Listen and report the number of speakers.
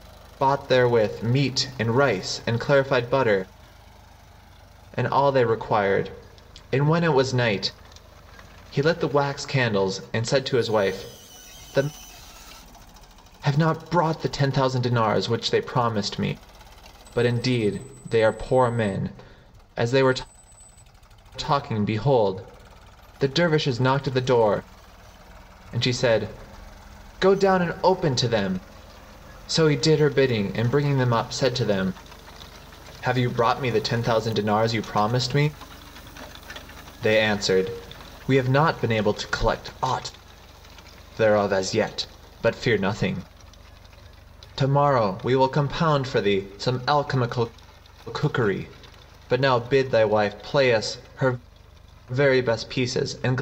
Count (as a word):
one